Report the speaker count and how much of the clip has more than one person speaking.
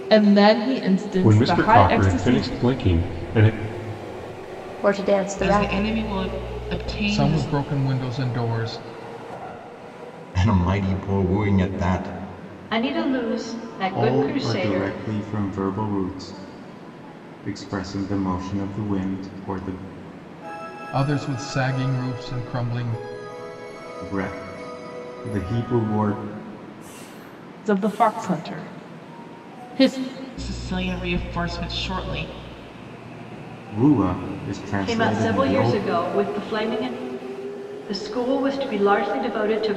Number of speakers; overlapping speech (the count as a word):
eight, about 11%